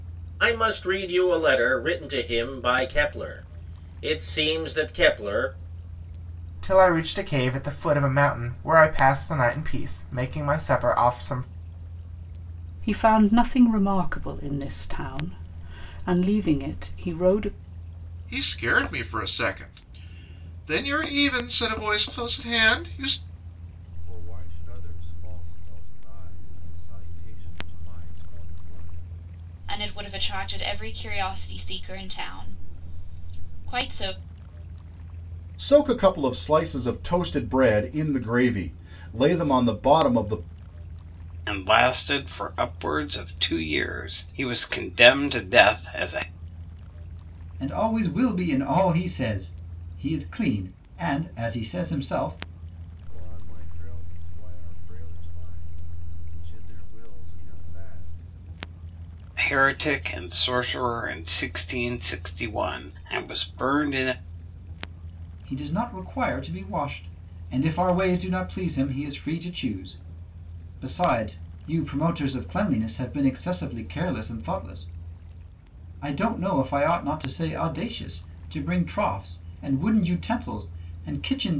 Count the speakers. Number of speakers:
nine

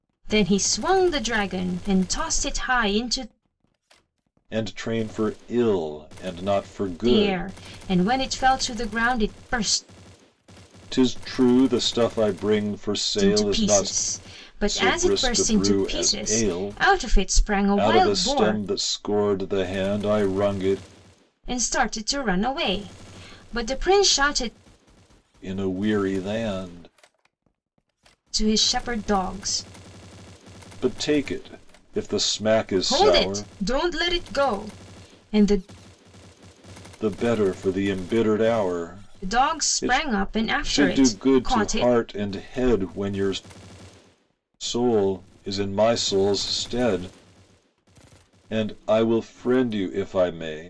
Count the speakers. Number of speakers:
two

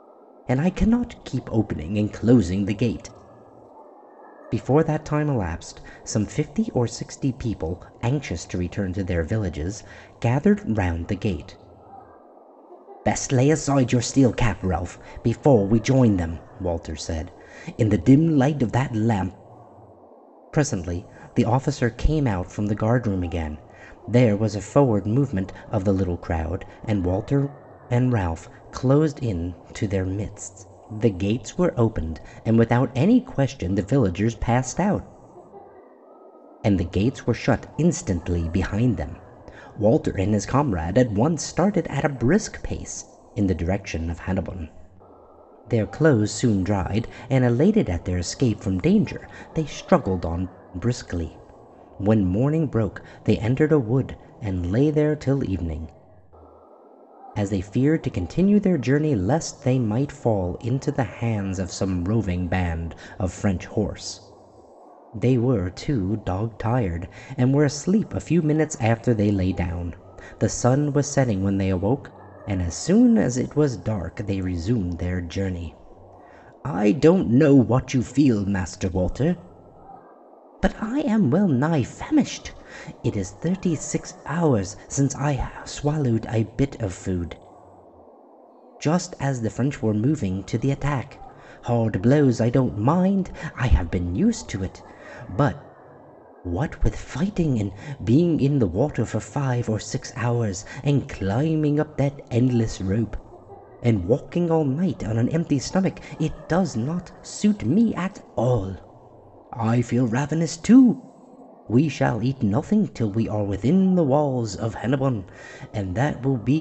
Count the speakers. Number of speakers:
one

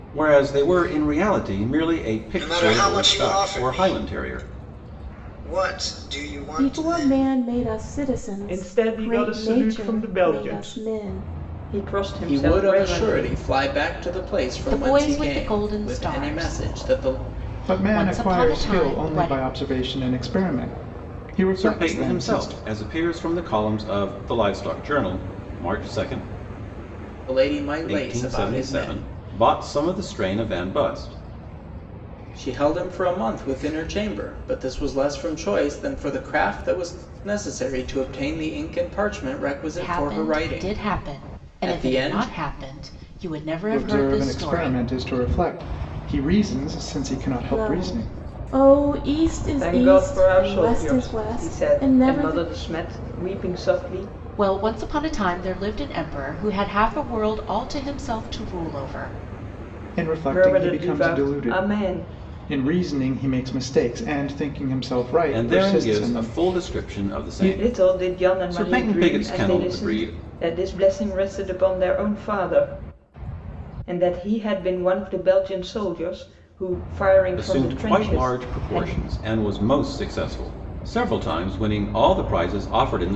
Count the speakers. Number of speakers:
seven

